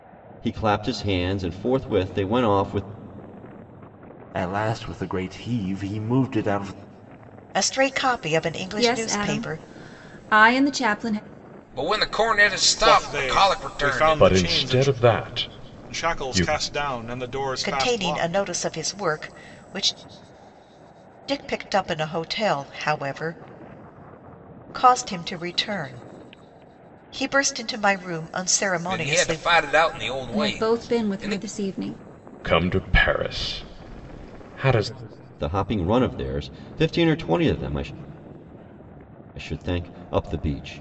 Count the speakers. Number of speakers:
seven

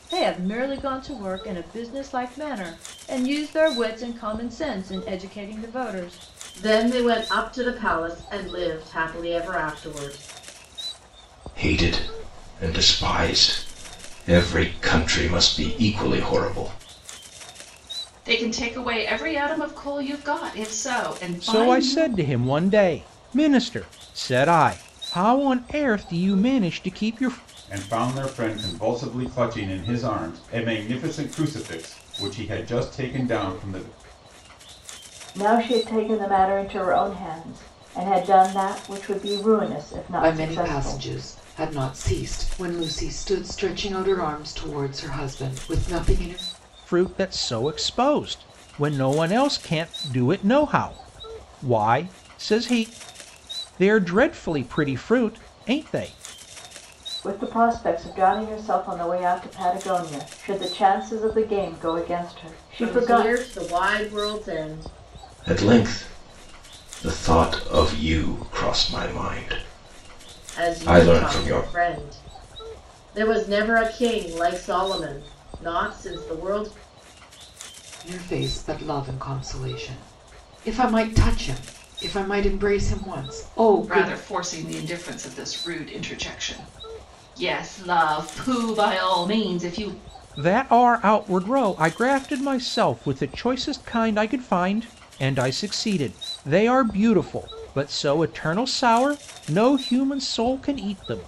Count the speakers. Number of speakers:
eight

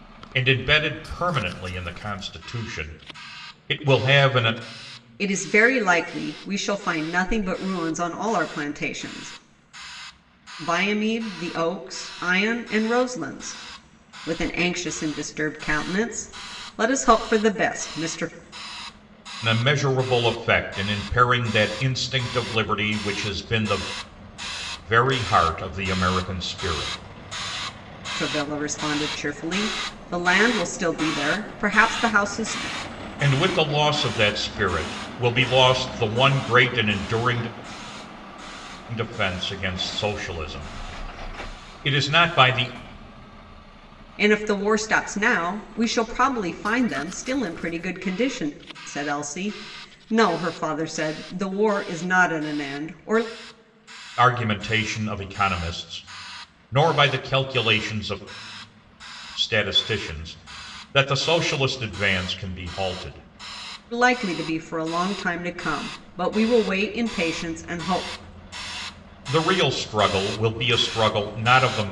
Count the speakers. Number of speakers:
two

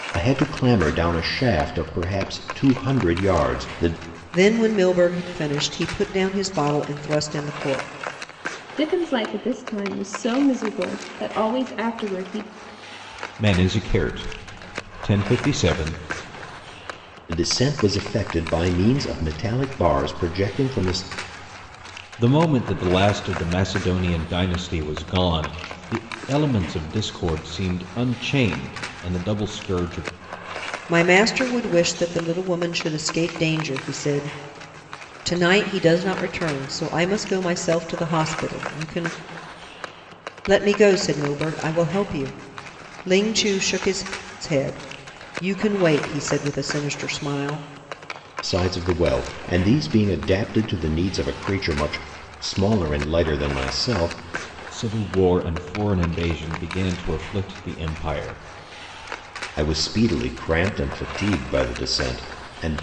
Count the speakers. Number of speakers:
four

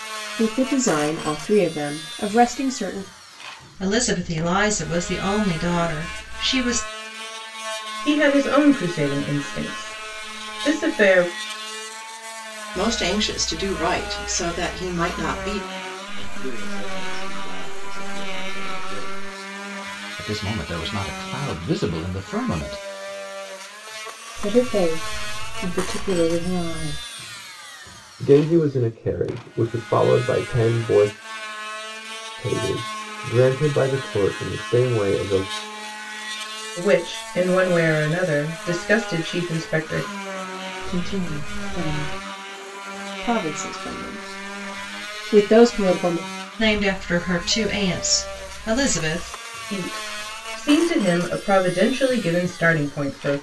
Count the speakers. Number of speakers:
eight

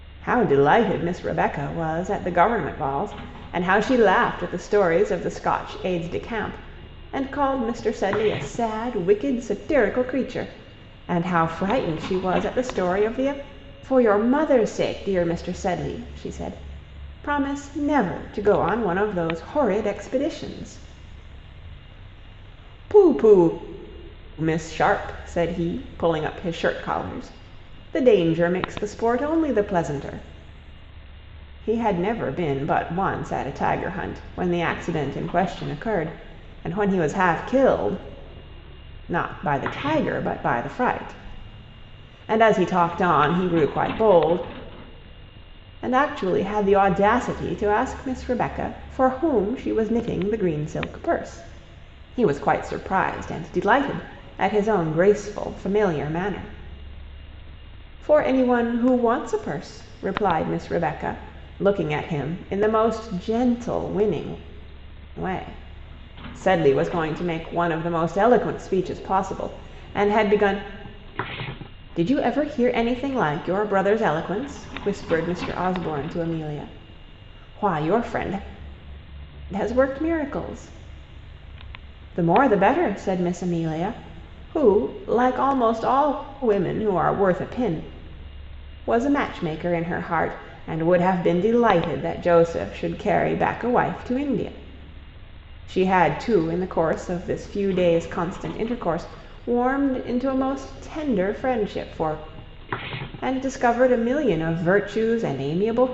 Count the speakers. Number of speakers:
one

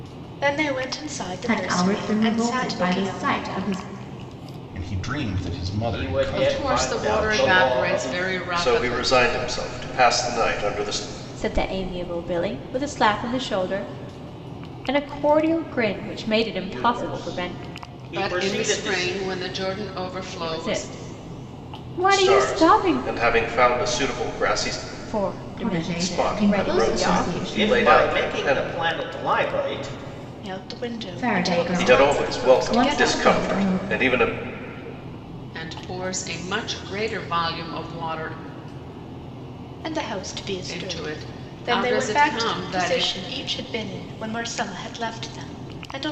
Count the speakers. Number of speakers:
seven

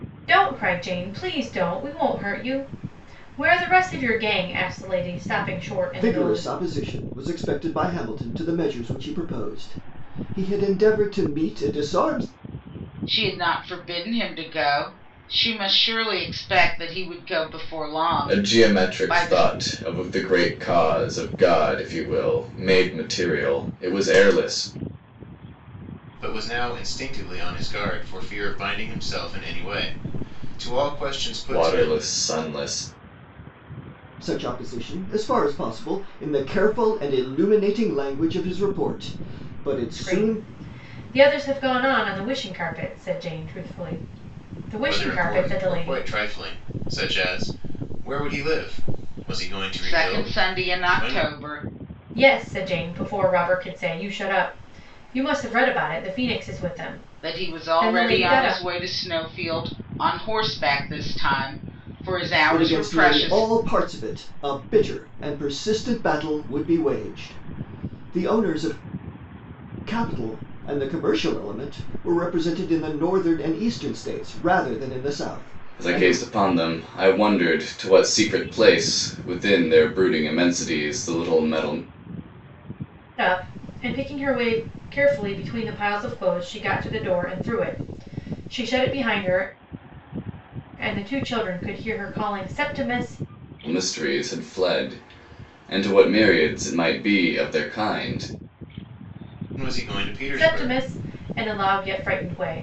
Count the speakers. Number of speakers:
five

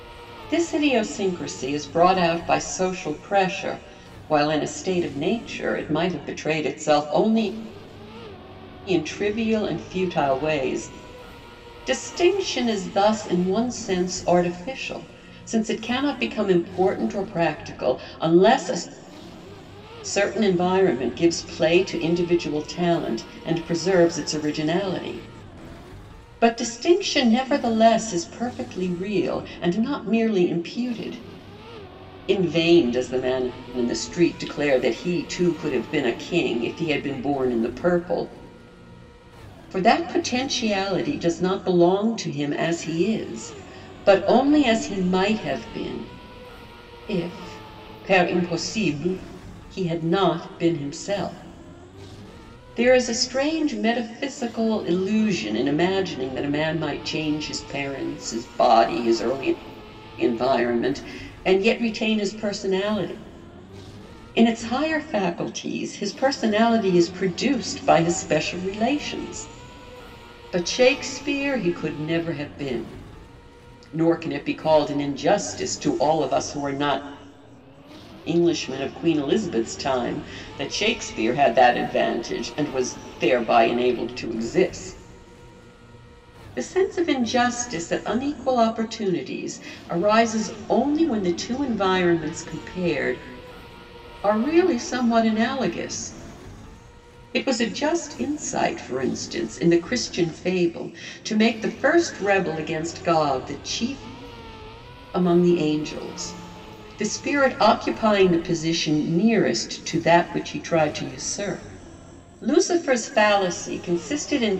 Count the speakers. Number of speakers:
one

